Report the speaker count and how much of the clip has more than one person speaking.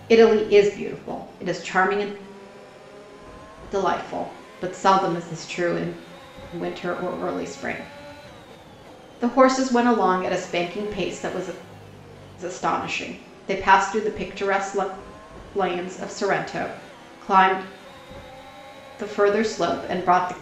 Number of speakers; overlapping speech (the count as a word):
one, no overlap